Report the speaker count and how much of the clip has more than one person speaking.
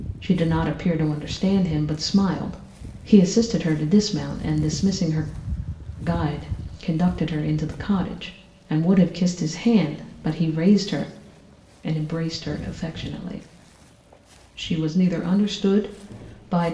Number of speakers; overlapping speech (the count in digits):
1, no overlap